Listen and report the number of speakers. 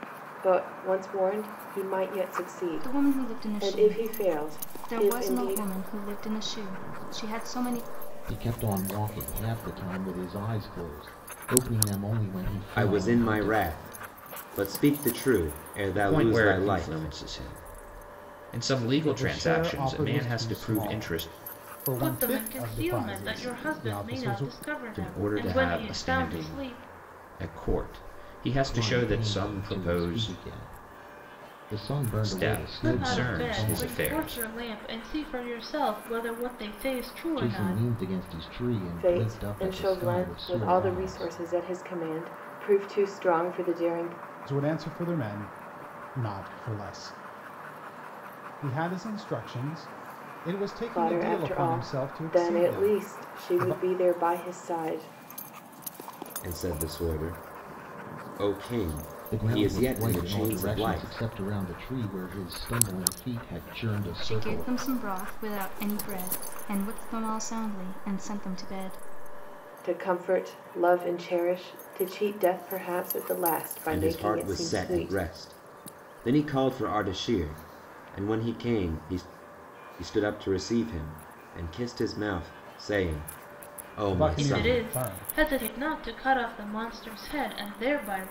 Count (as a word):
seven